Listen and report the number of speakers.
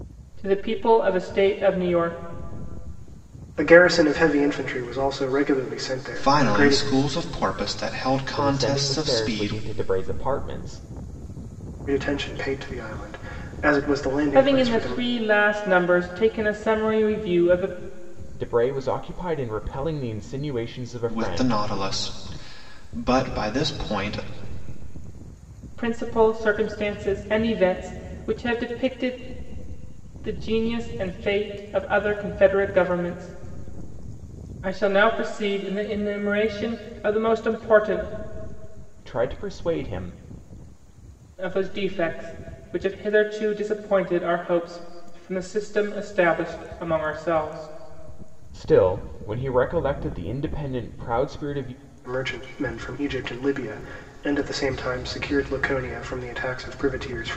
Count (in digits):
4